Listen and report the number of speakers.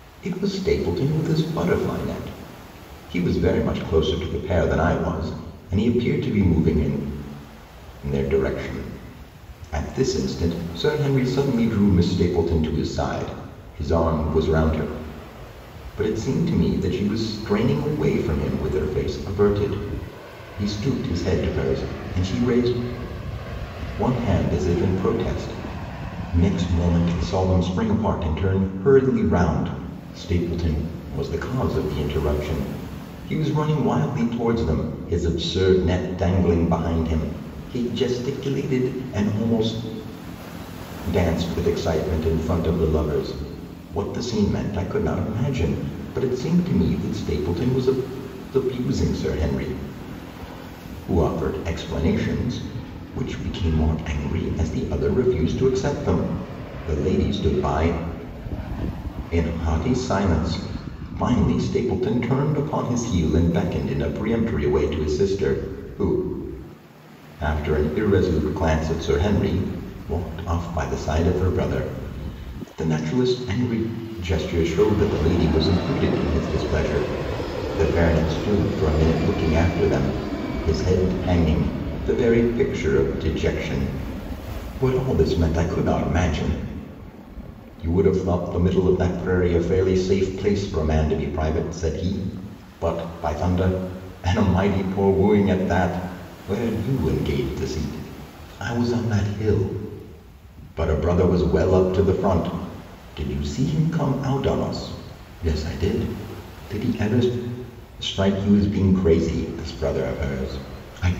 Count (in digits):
1